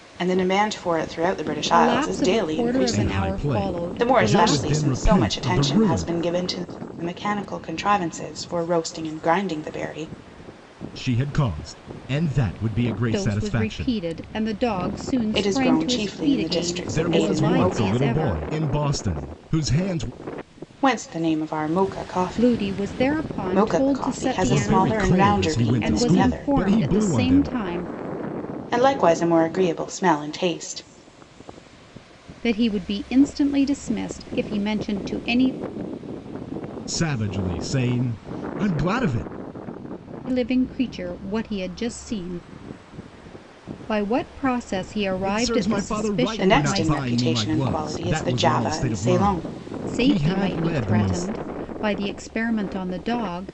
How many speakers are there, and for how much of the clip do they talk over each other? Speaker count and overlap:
3, about 36%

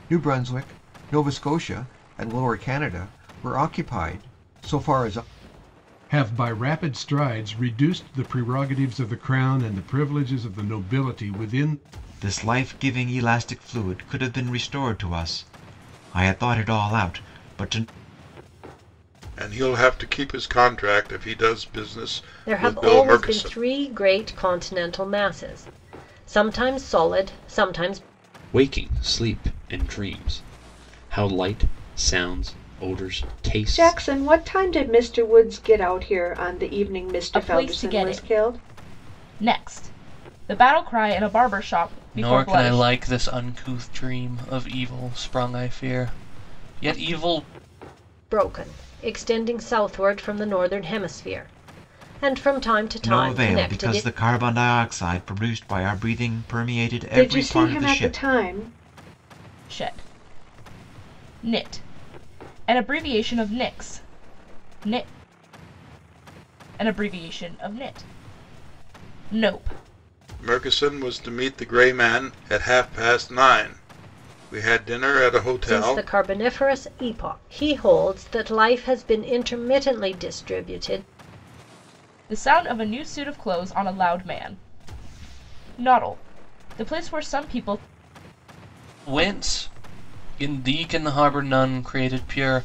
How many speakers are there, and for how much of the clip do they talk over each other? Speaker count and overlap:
9, about 7%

